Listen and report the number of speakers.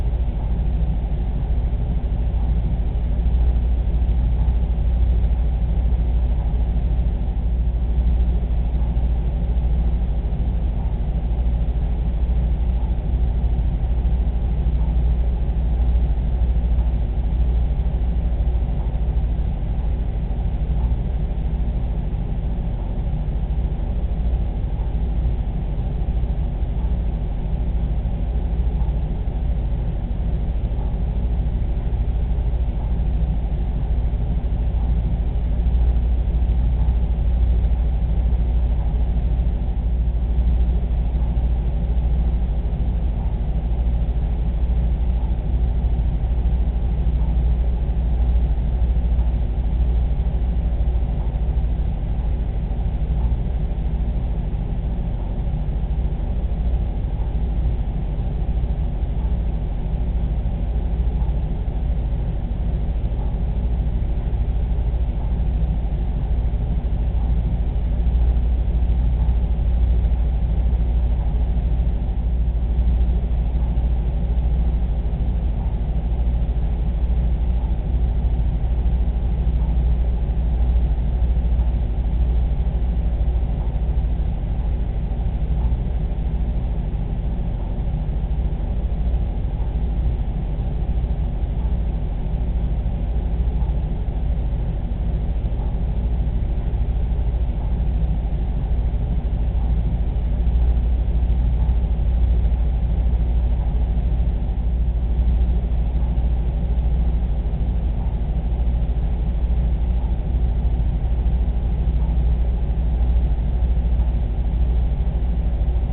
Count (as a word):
zero